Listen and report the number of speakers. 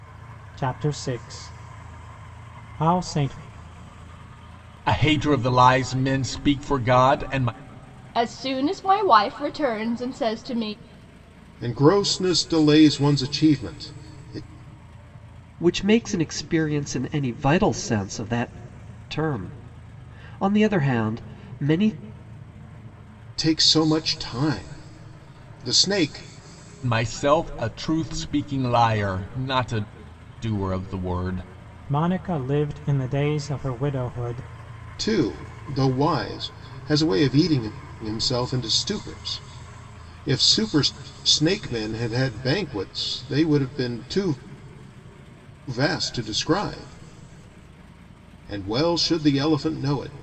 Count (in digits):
5